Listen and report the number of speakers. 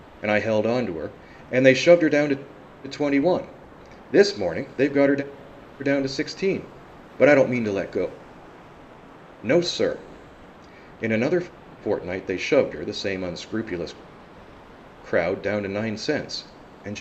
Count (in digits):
1